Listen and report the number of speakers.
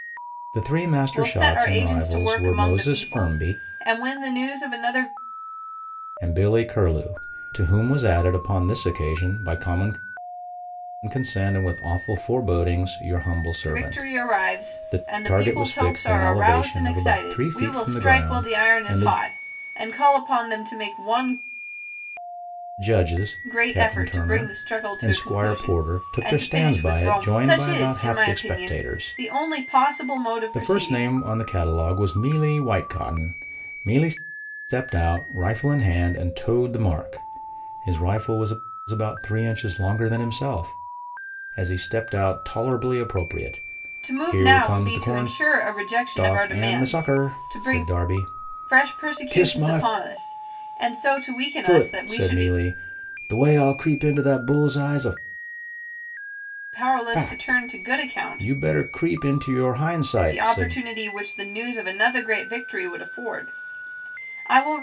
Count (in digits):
2